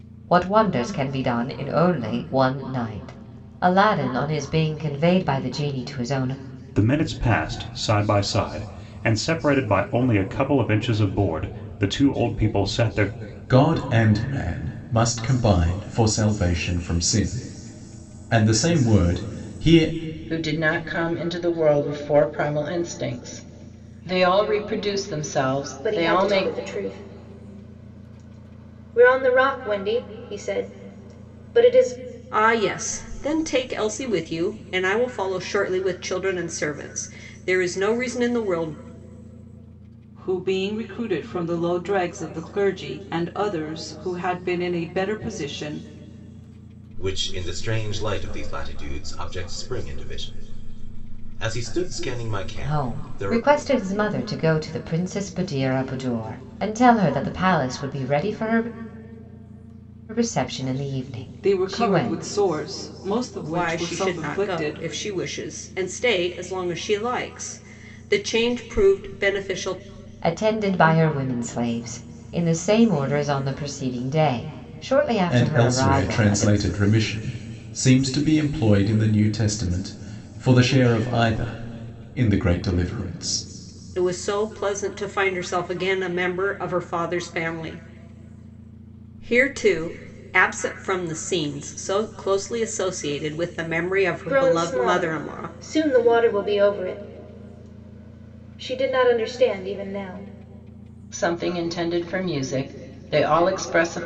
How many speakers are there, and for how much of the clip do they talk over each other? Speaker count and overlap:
8, about 6%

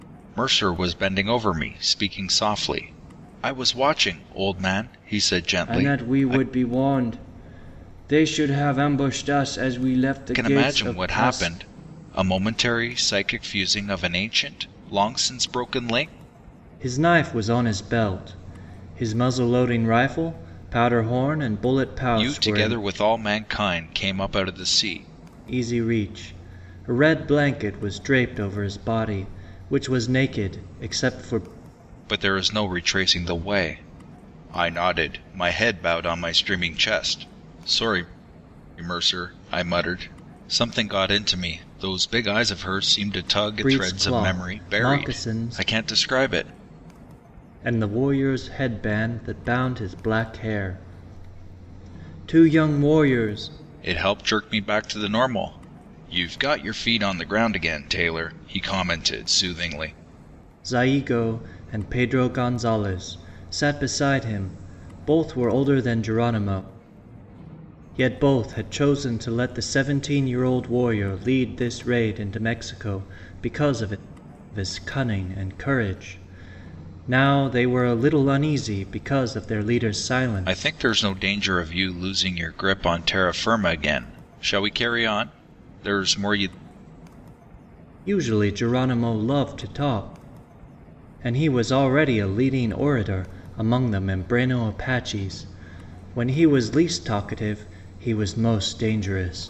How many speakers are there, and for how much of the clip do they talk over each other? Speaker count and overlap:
2, about 5%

